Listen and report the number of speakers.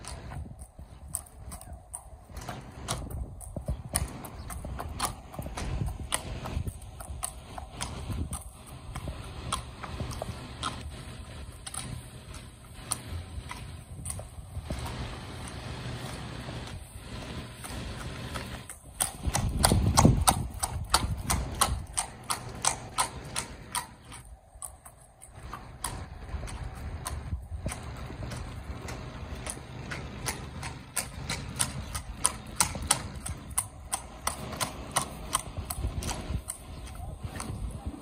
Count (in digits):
0